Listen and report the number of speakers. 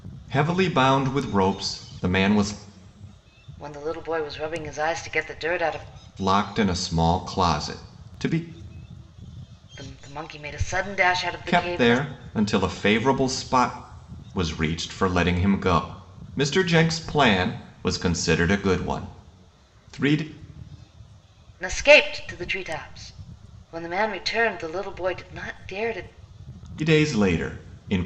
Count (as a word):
two